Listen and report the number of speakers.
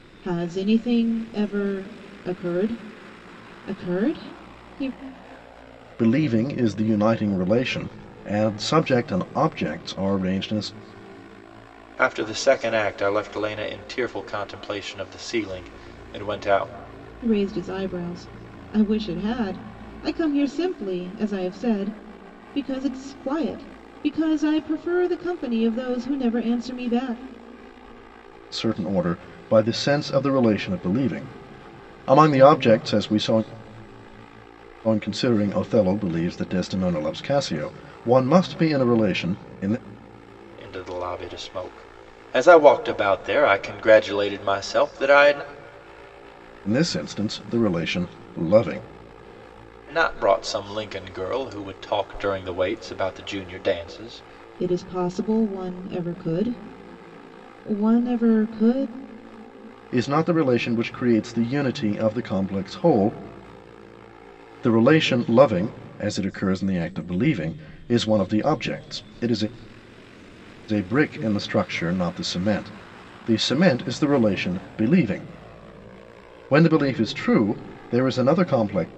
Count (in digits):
3